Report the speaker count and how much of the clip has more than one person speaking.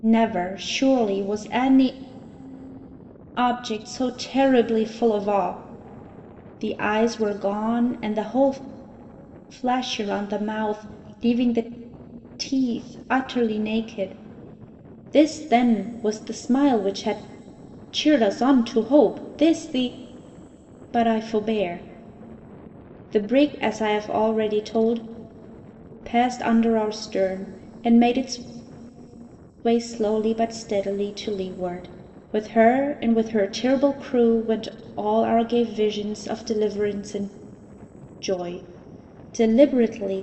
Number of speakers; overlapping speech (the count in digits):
1, no overlap